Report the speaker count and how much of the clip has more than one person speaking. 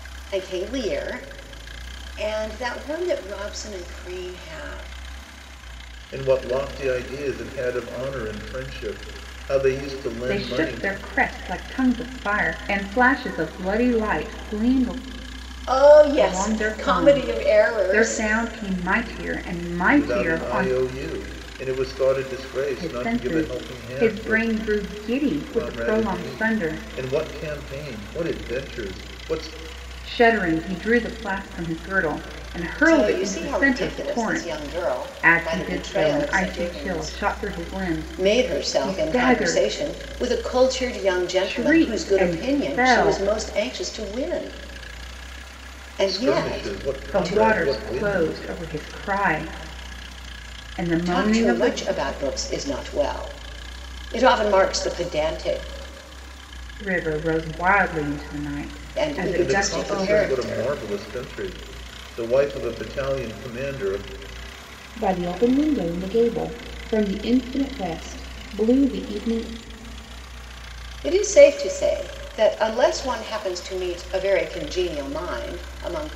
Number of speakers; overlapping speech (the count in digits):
3, about 24%